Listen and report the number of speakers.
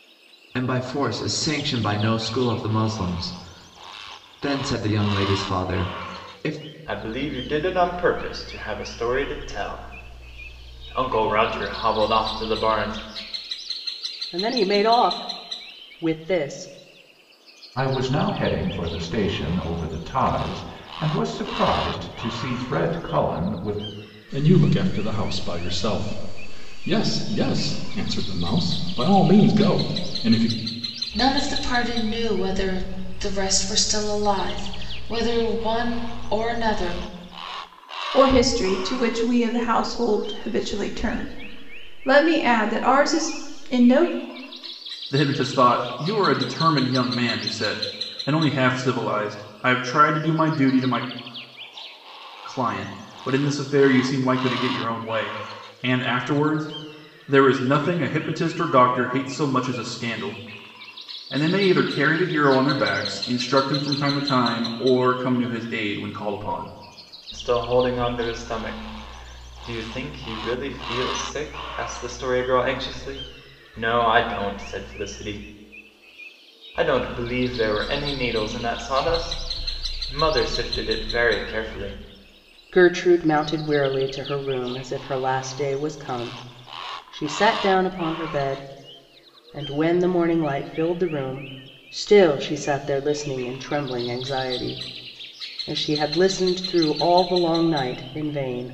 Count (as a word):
eight